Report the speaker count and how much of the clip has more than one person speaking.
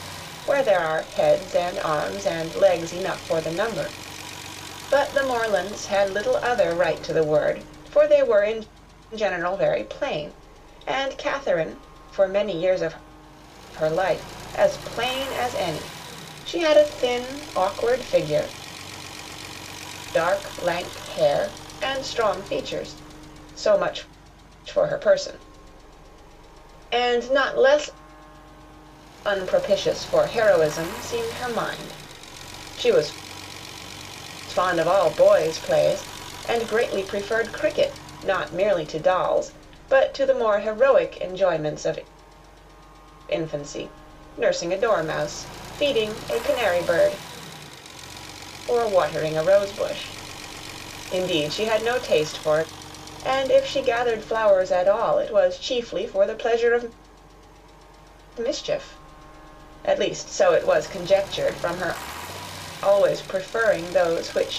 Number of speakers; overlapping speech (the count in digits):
1, no overlap